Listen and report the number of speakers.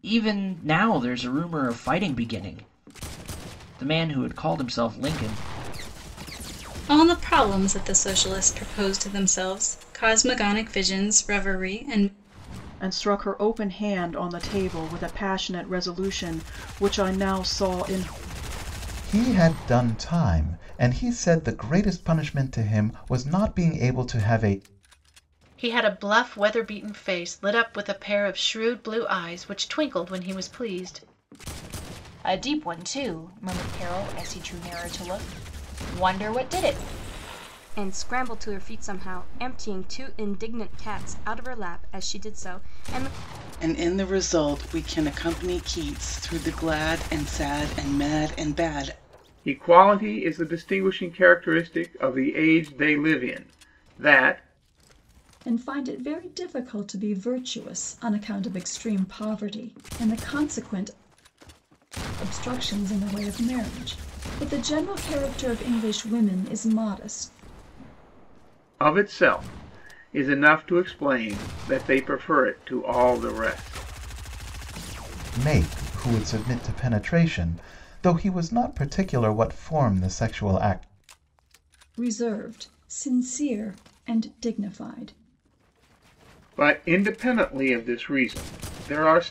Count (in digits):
10